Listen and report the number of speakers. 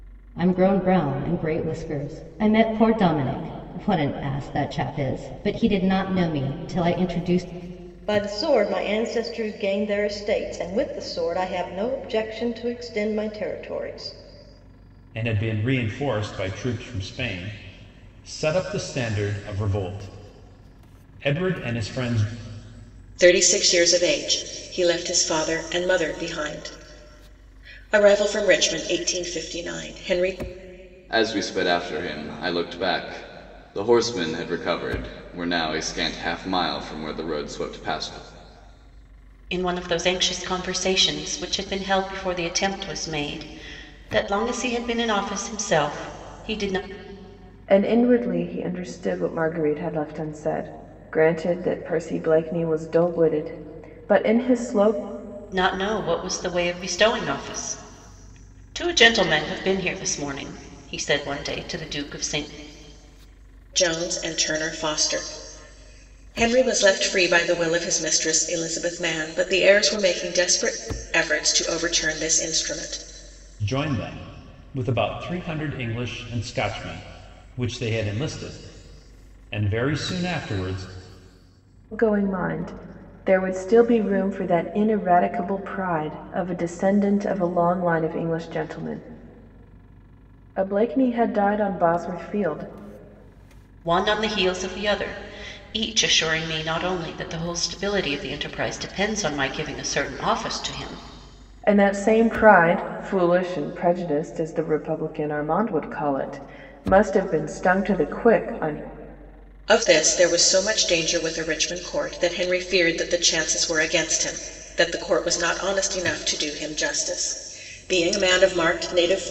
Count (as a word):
seven